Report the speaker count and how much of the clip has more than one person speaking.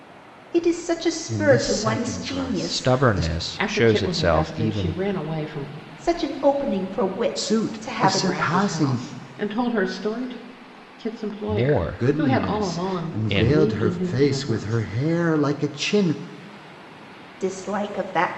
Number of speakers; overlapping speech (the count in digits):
4, about 46%